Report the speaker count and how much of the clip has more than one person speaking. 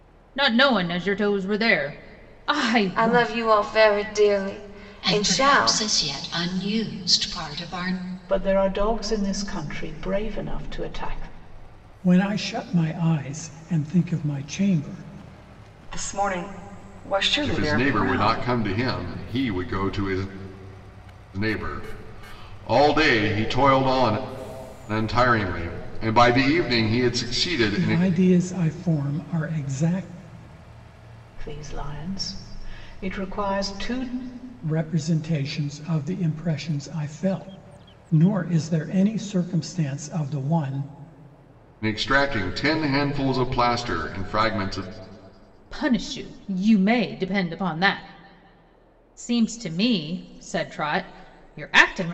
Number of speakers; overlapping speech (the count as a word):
seven, about 5%